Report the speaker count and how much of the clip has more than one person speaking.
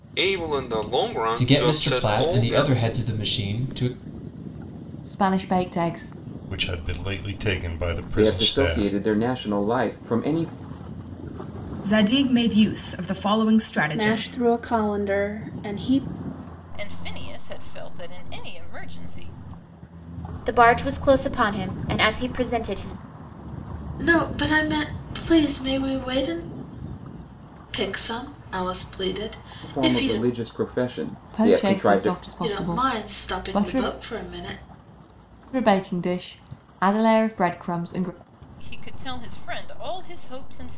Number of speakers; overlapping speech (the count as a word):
ten, about 14%